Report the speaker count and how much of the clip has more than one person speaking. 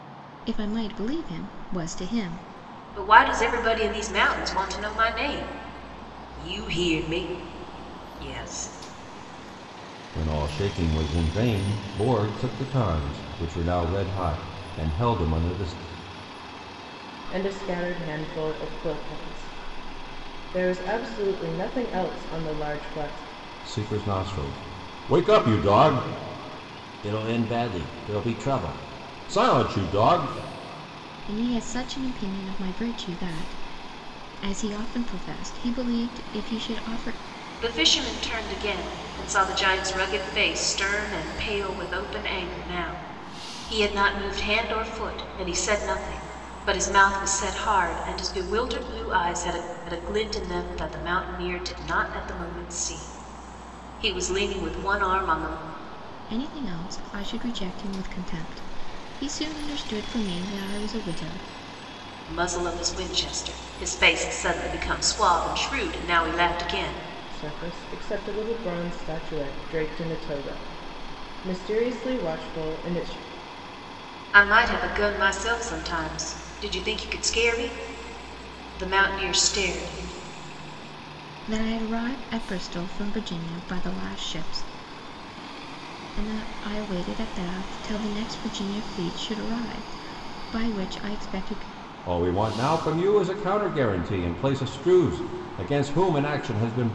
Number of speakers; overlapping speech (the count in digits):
4, no overlap